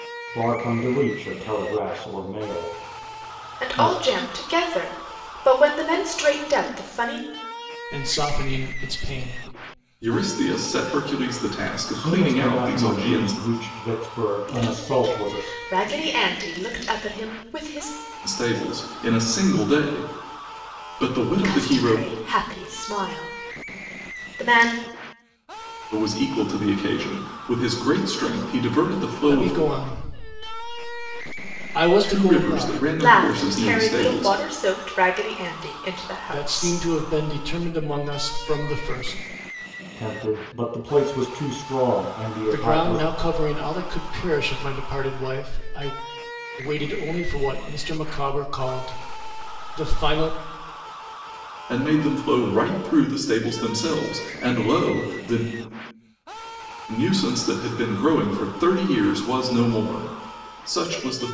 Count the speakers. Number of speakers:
4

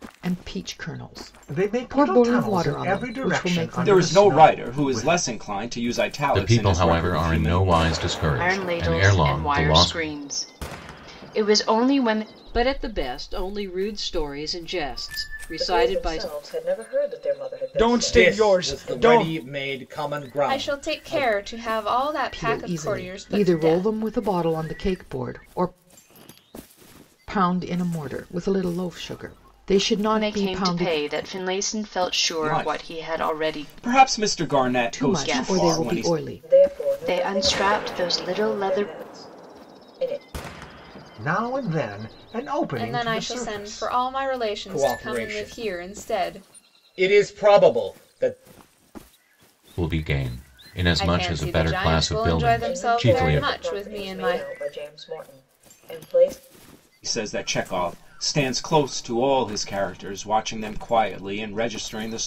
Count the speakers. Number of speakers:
10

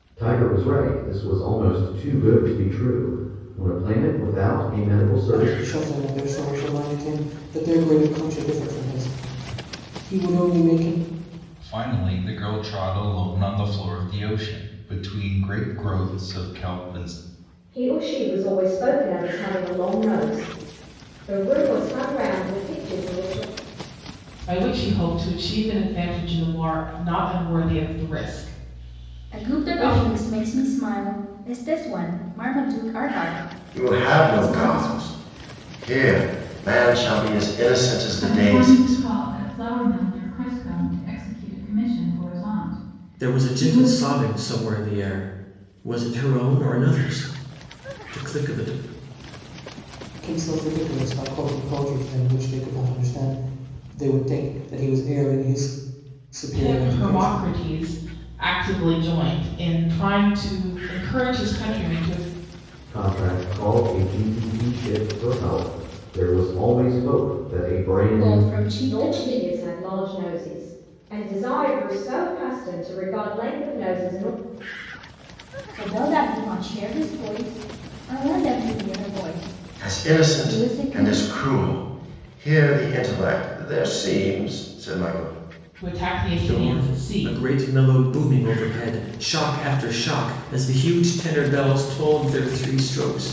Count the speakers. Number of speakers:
9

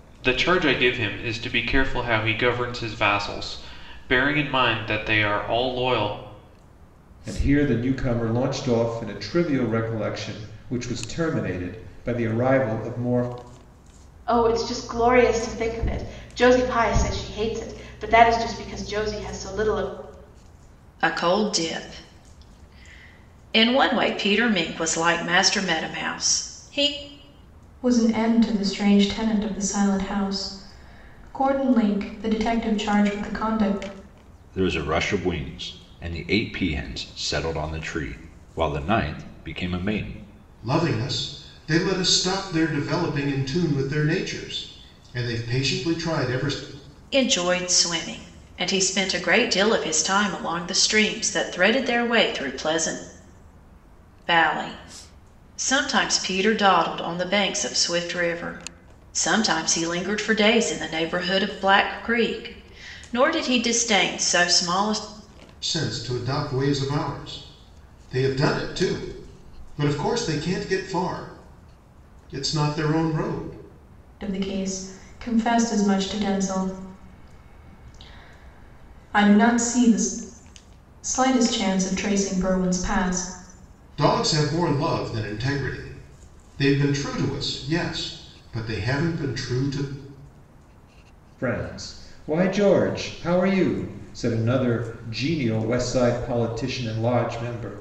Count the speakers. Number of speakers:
7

